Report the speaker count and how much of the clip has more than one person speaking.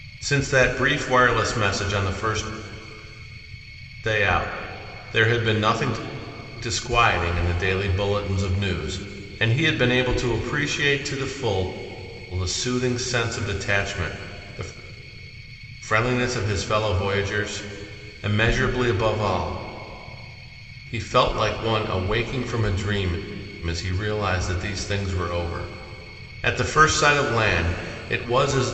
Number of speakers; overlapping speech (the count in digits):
1, no overlap